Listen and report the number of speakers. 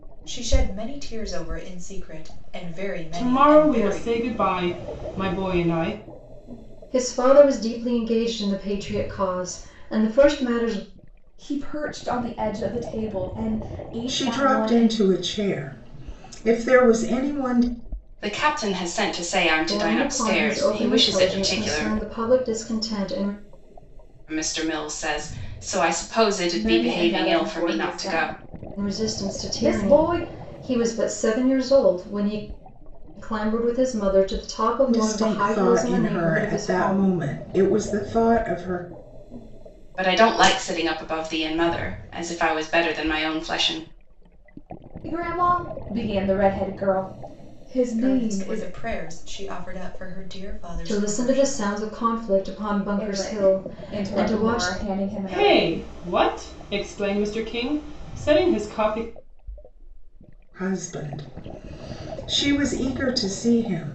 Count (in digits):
6